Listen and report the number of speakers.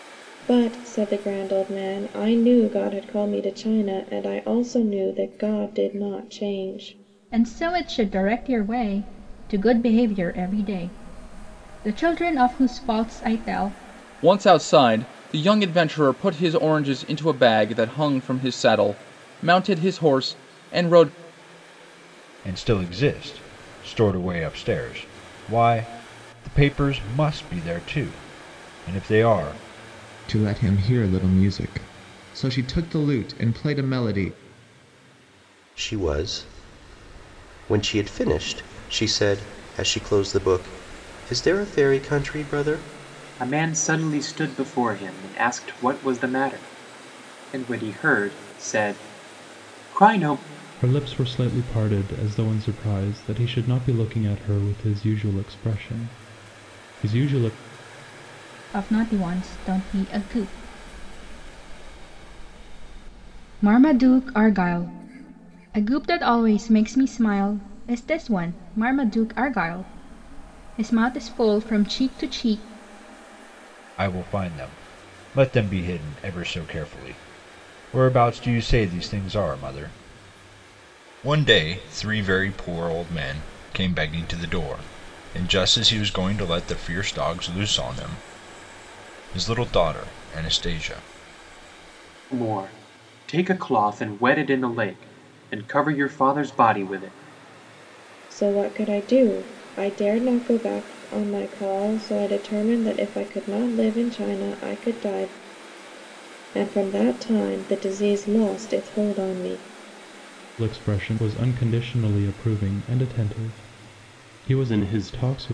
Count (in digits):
8